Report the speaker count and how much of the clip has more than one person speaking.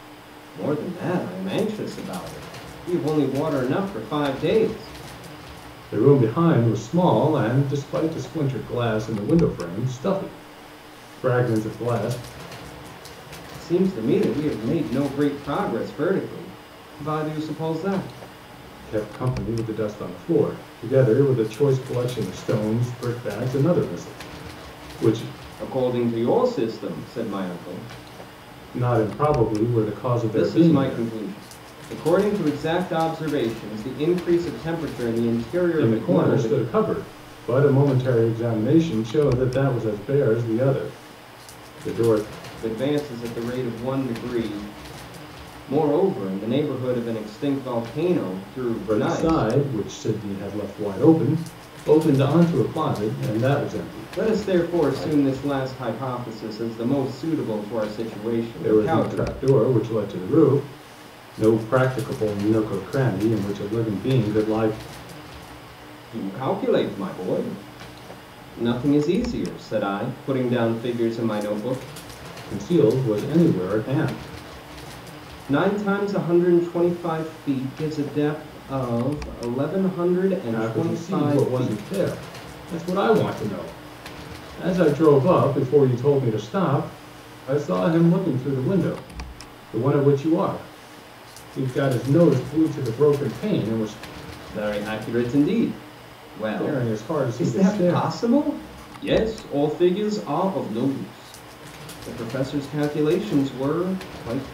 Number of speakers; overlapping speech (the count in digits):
2, about 7%